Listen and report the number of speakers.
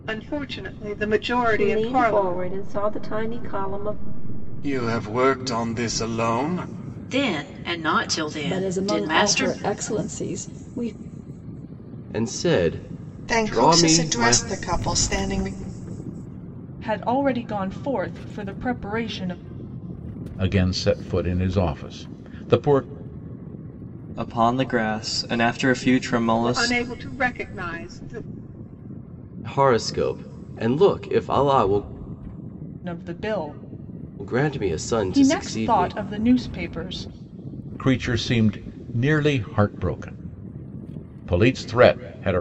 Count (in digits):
10